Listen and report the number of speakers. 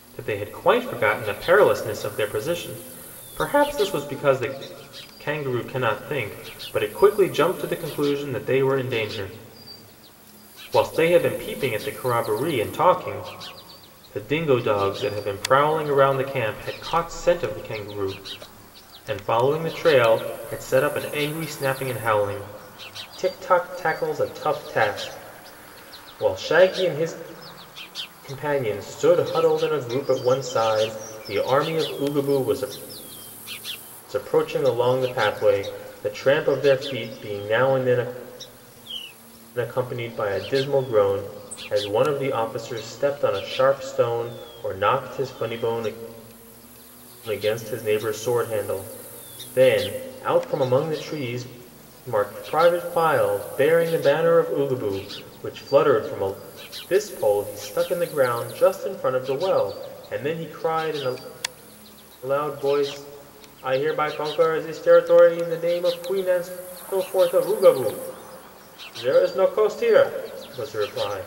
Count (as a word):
one